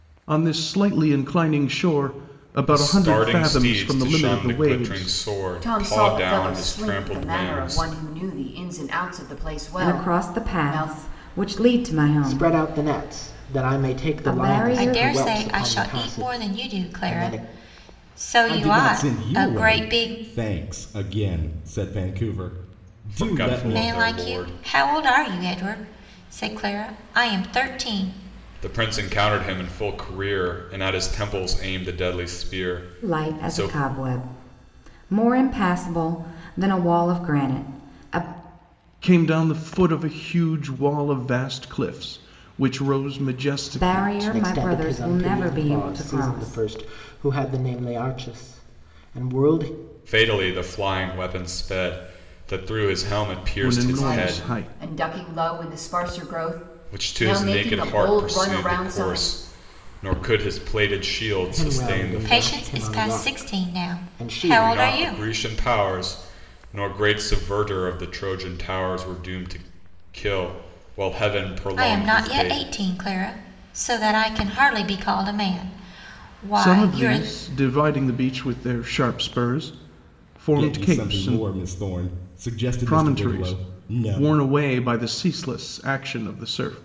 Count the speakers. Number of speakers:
seven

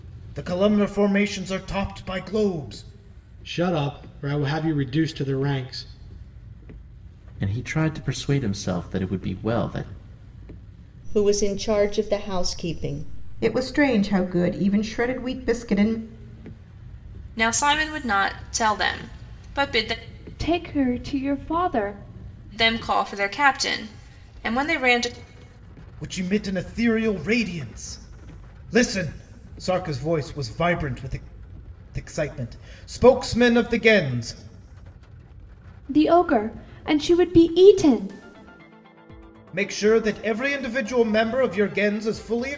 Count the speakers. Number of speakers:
seven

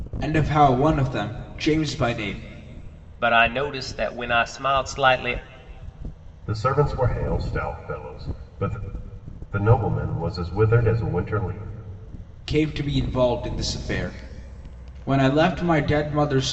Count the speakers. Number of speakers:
three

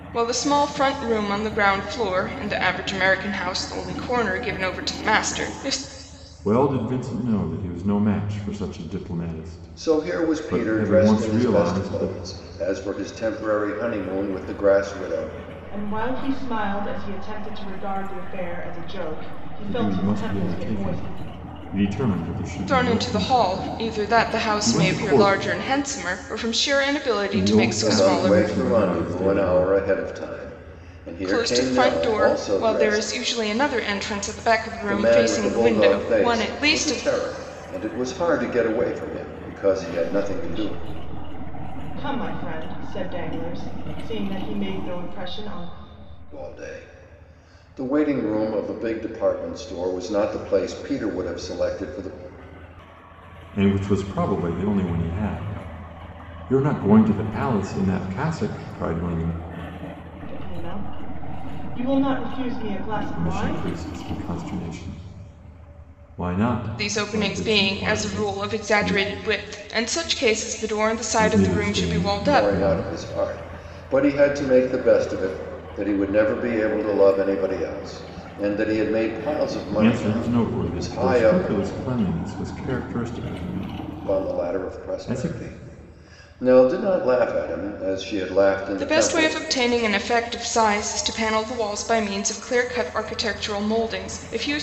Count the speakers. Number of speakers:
four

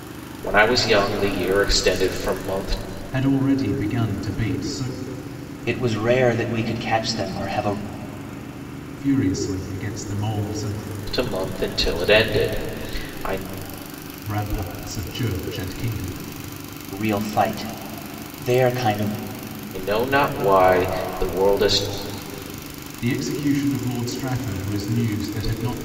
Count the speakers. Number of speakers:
three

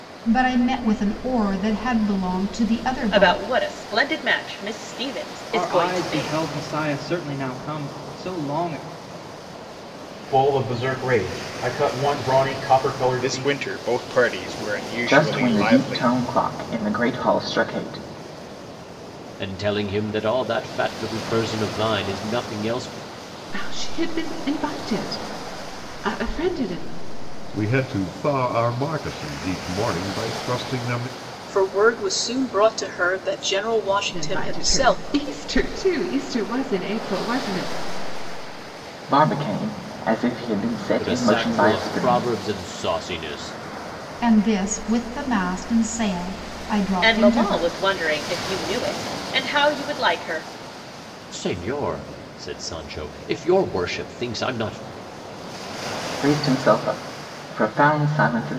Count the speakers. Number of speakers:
ten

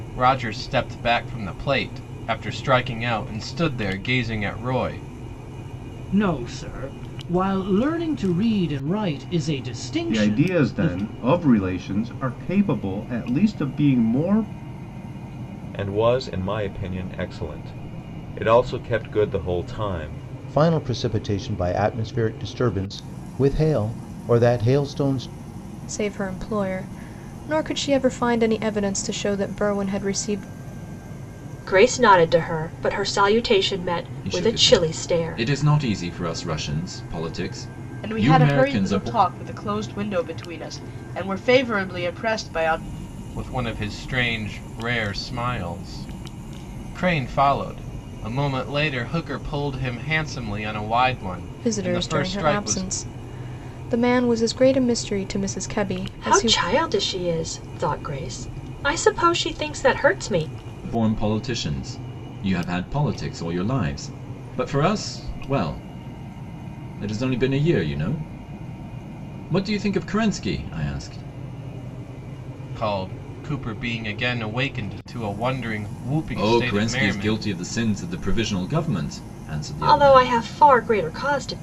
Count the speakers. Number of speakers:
nine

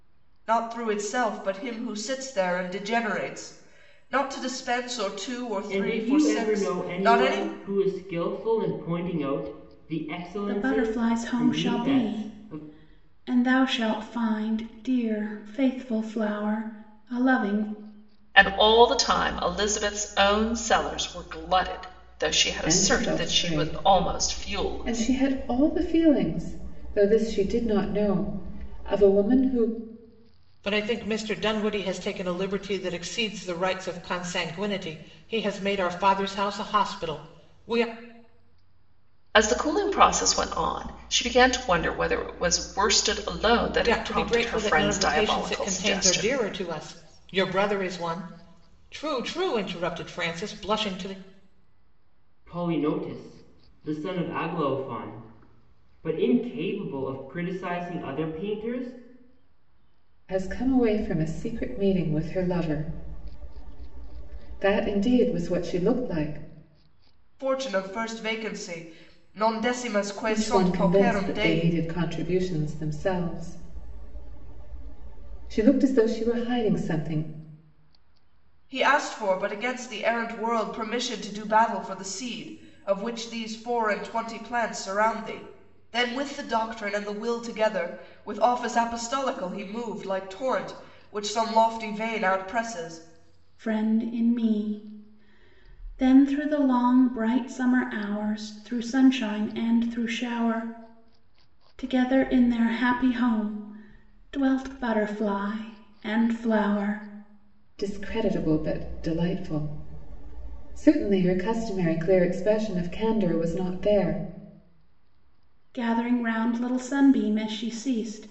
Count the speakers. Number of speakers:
six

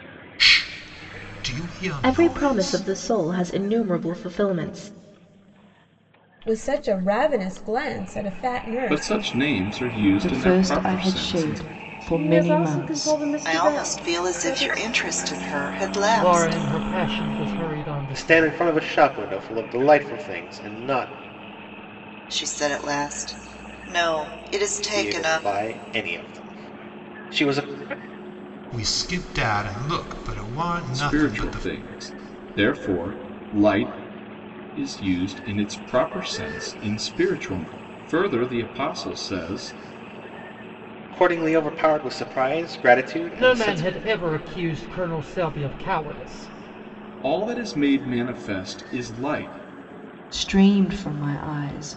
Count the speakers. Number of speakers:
nine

